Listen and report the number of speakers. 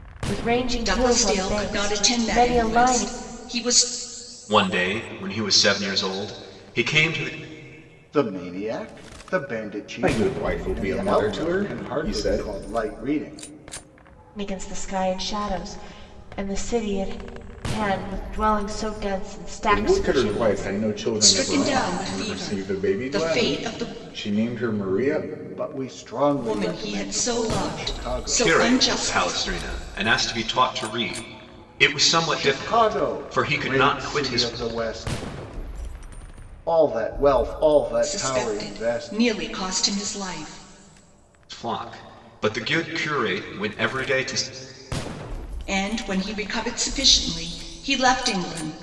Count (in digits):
5